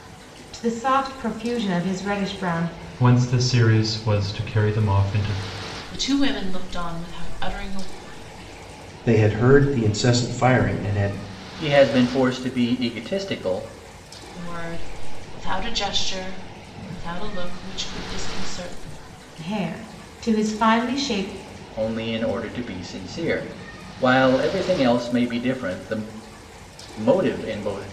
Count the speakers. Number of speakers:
5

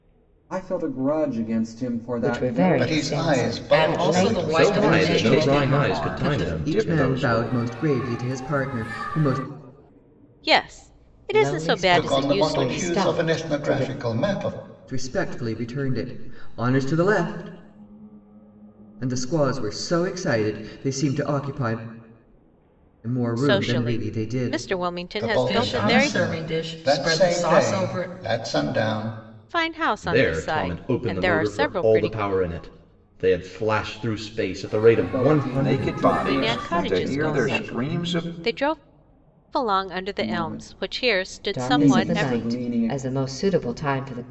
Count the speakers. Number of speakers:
8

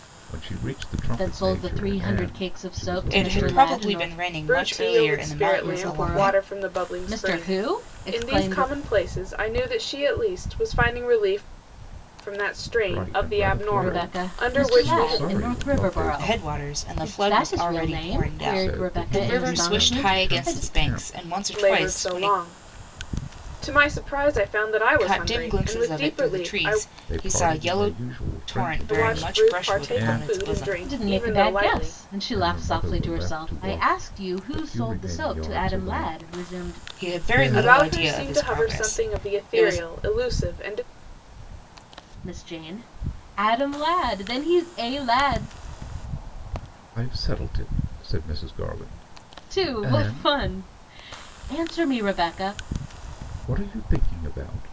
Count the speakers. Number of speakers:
4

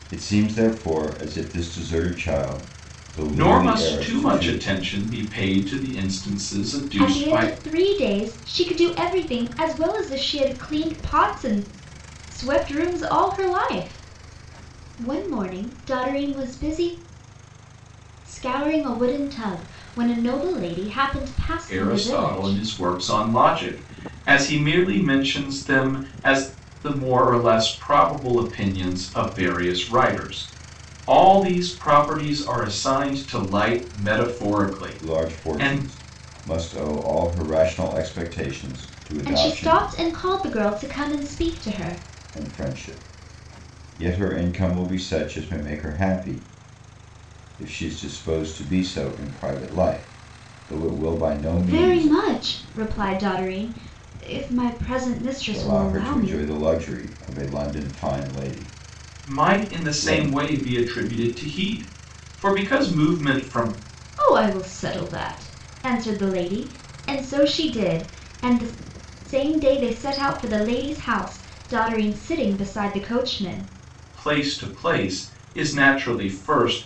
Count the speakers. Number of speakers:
3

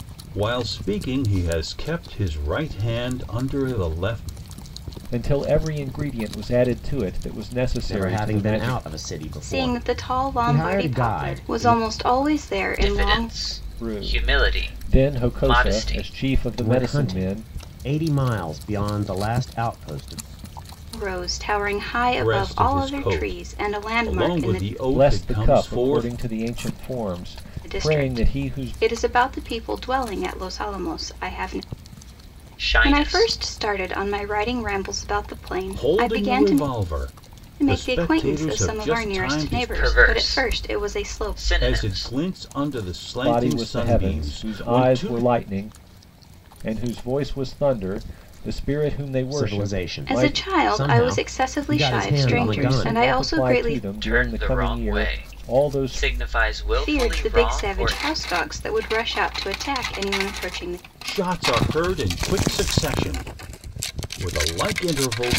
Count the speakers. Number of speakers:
5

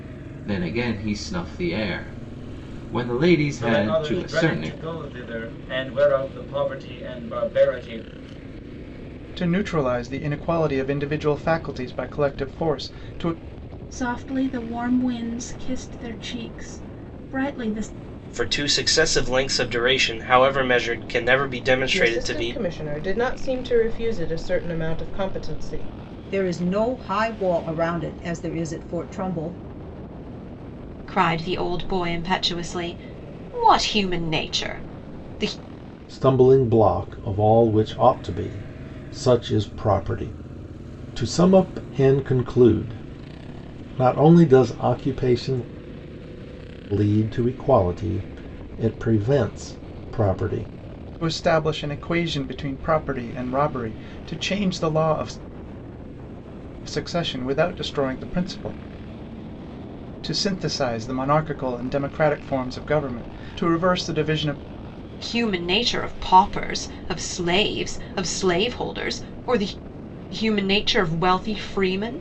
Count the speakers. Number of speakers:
9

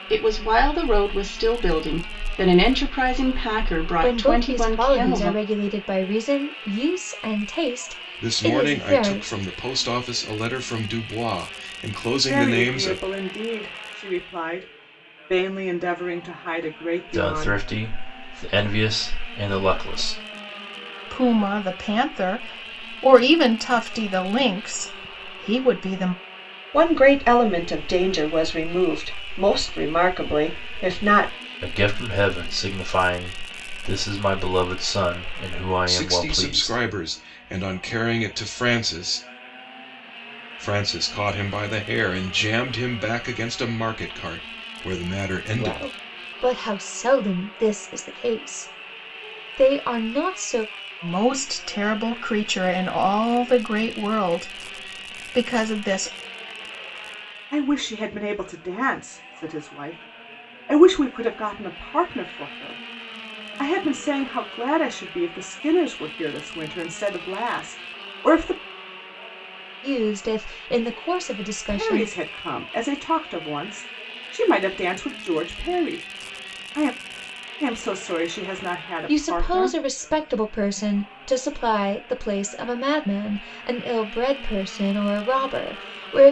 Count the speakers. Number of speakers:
7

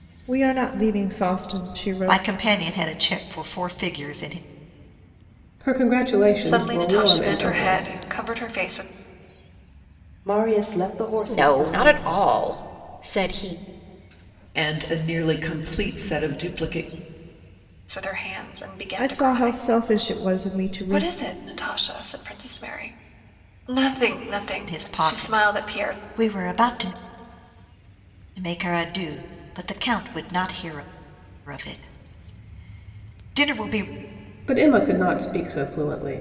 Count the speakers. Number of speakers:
7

